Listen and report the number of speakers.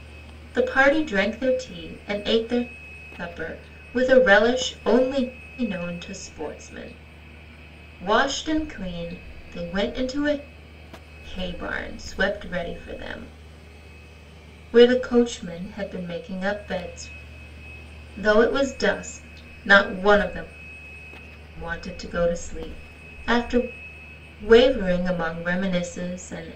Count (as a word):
one